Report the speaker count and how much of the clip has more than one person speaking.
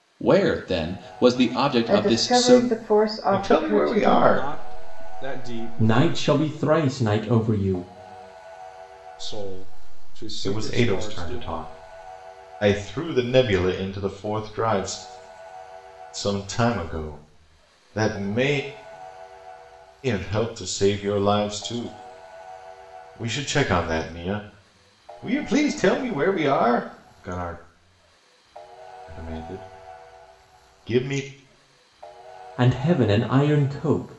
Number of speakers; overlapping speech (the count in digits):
5, about 10%